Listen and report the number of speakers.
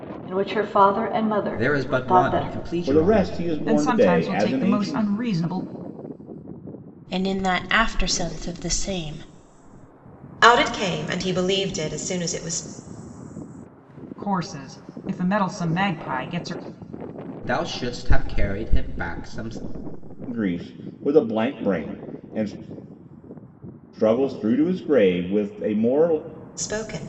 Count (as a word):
six